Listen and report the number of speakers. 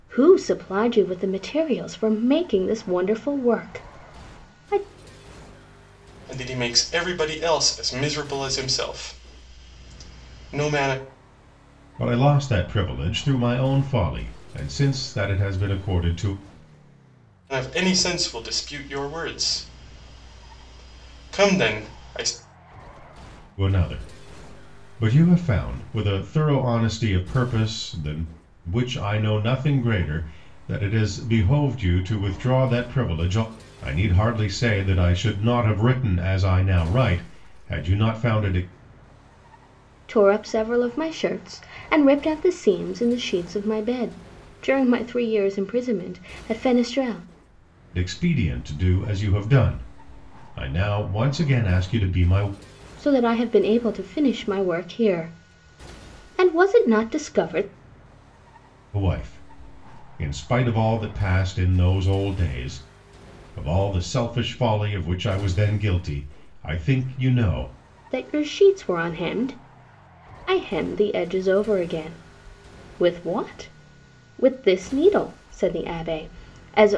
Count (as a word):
three